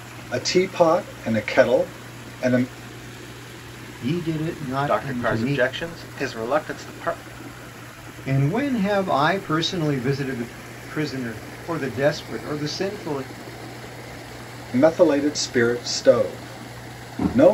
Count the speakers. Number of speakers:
3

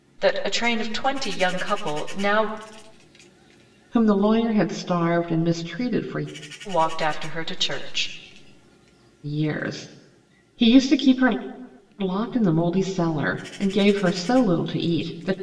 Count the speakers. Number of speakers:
2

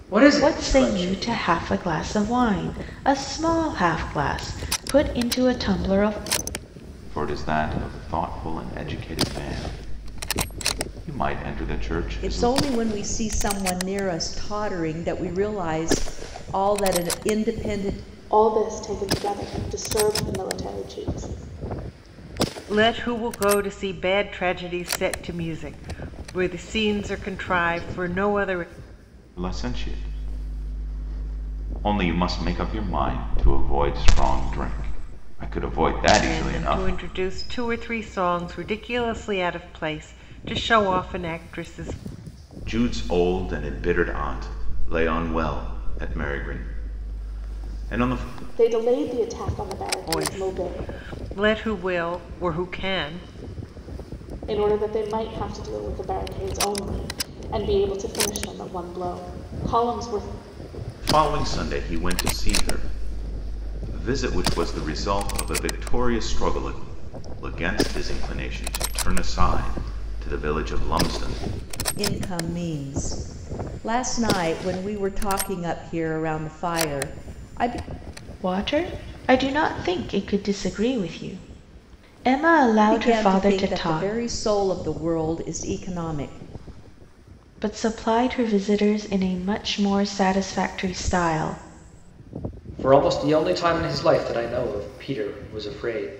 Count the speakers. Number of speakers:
6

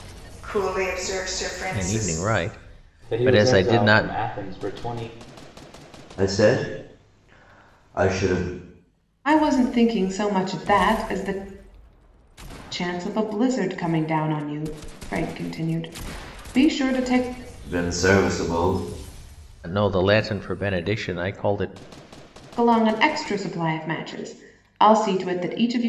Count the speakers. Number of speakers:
5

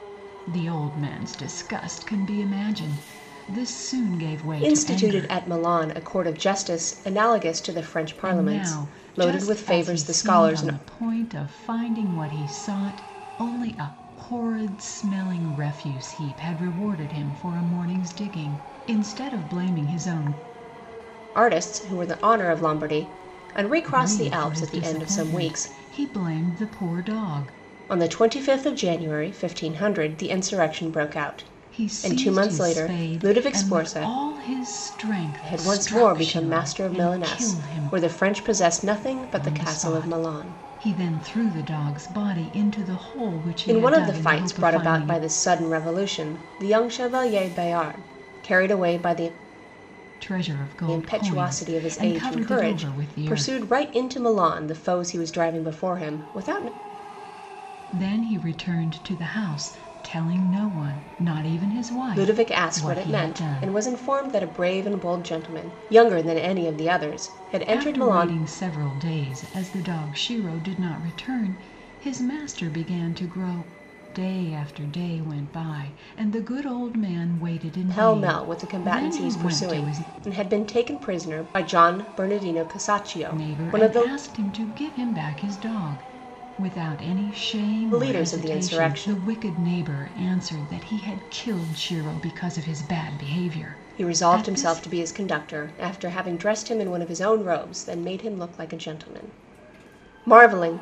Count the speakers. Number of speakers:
2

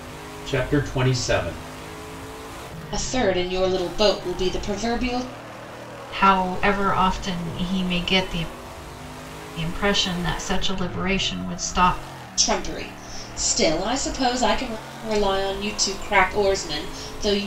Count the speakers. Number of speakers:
3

